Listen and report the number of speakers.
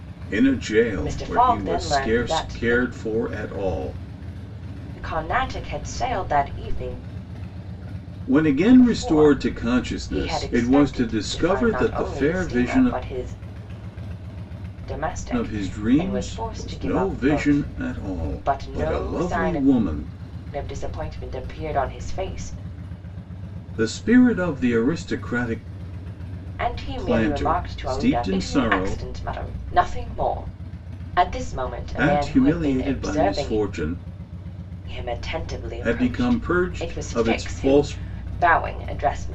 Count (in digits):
2